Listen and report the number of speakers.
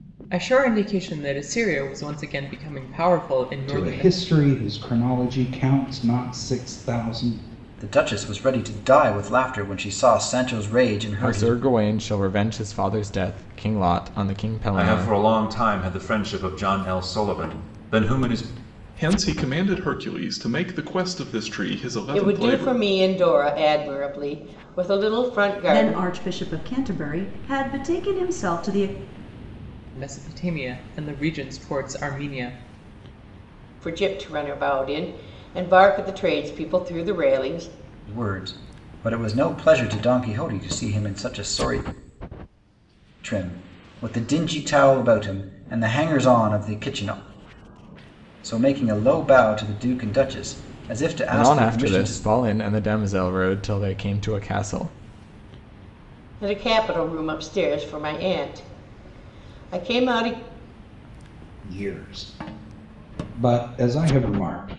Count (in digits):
8